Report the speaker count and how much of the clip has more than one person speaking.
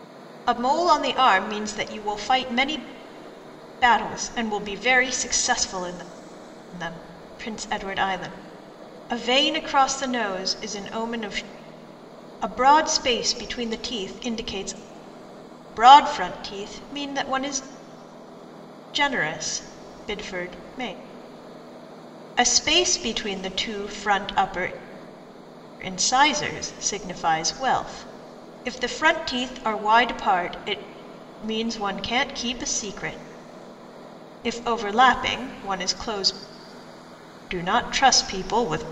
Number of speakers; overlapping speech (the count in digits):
1, no overlap